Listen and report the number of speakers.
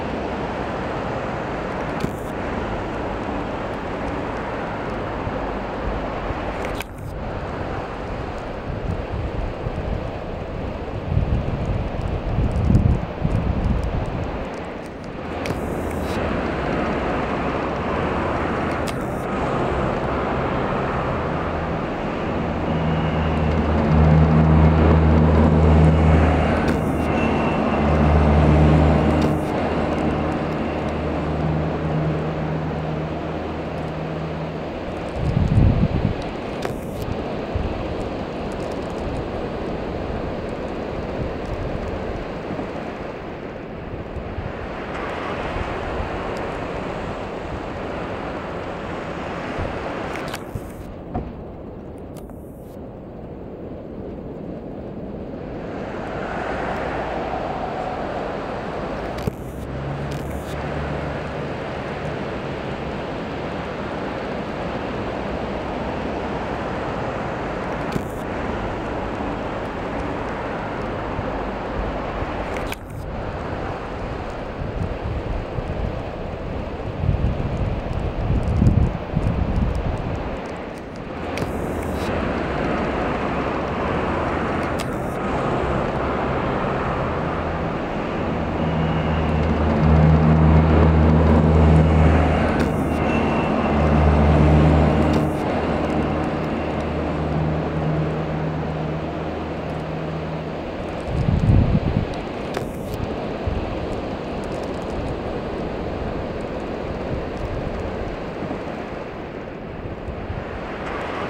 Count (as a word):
zero